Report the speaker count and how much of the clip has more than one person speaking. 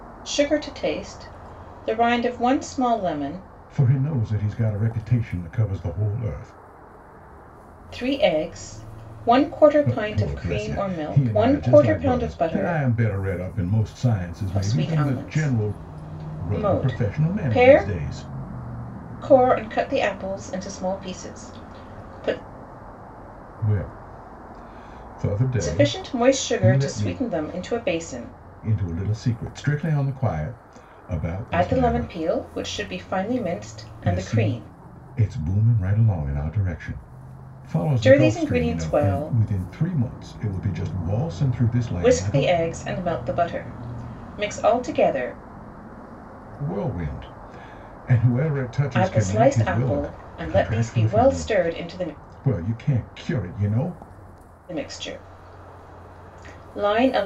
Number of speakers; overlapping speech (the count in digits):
2, about 24%